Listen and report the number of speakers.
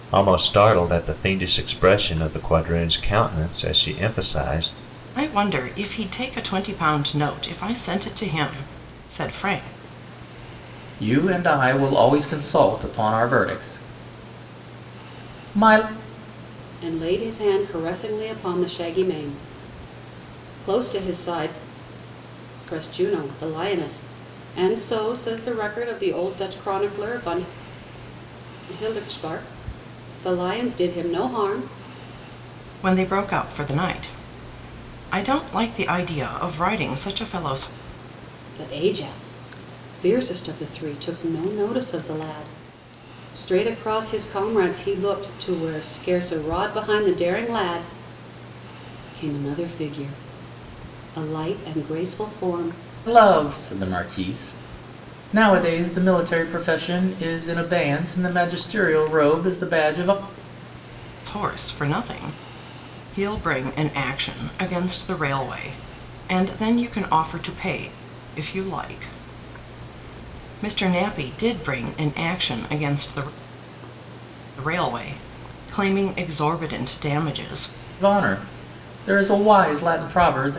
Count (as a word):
four